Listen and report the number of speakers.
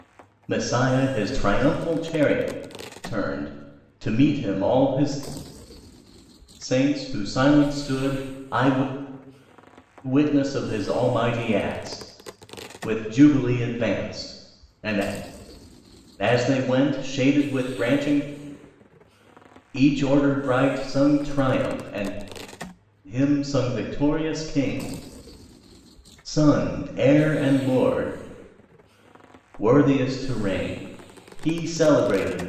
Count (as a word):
one